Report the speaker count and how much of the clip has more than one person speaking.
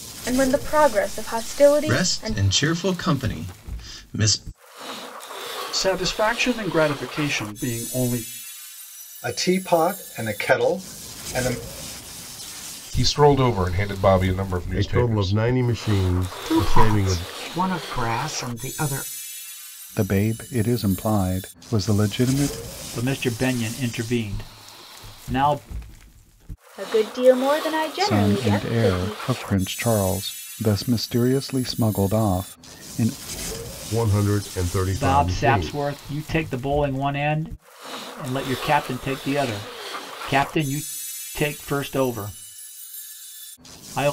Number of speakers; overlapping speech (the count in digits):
10, about 10%